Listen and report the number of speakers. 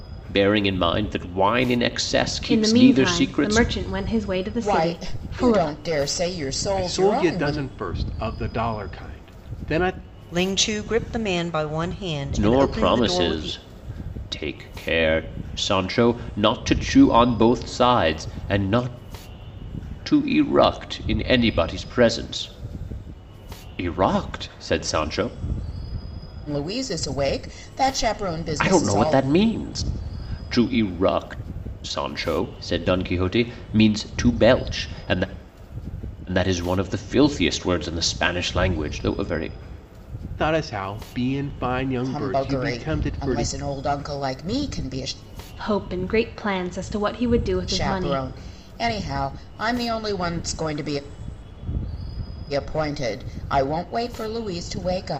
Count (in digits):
5